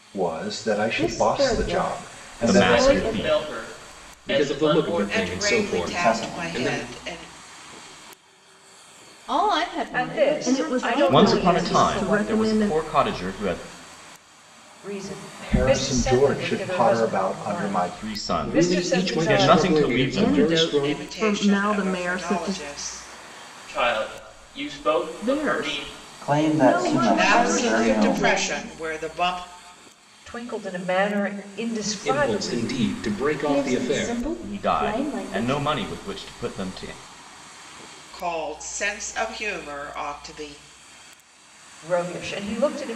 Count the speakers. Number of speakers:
10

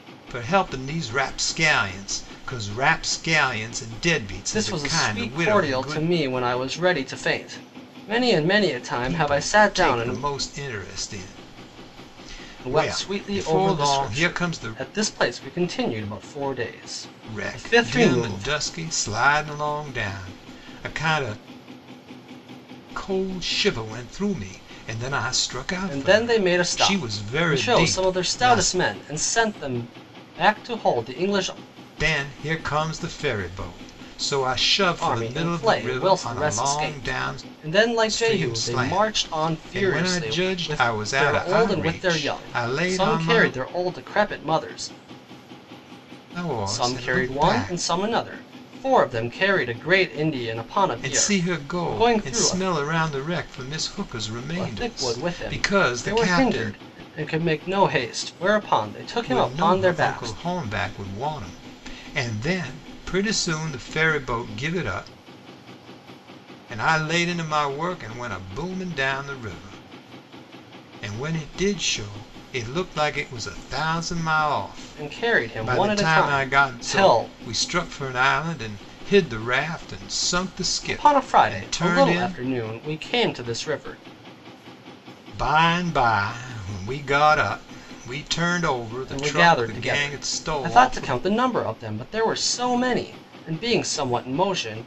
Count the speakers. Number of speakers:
2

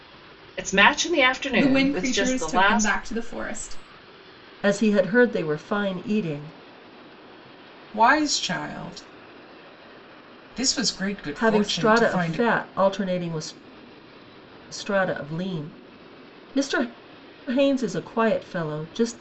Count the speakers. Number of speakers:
4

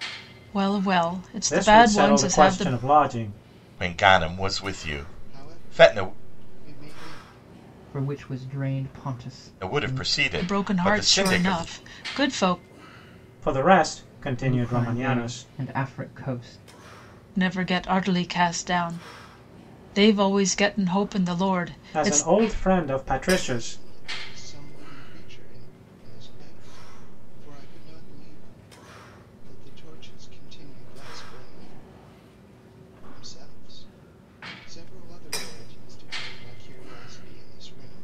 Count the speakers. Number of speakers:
5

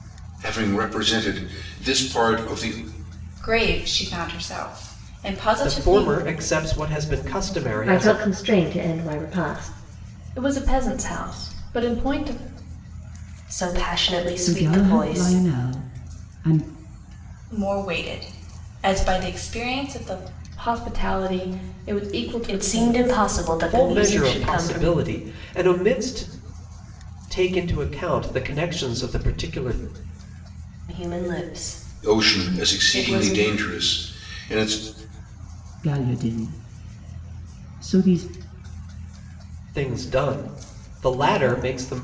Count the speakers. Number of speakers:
7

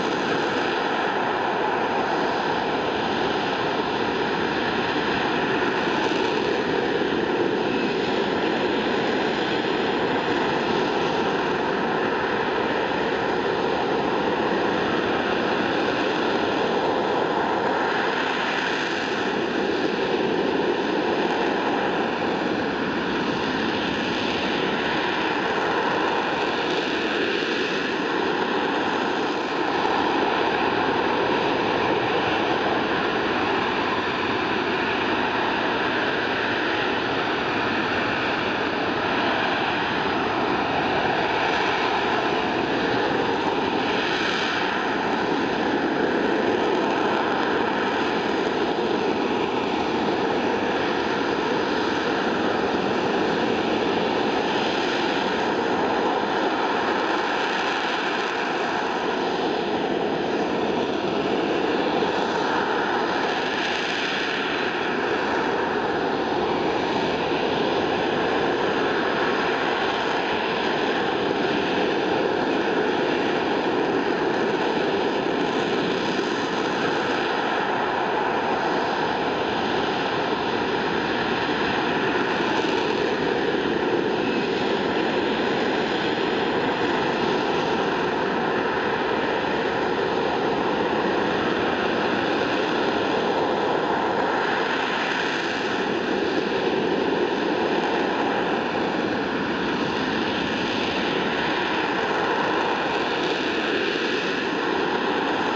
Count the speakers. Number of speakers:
0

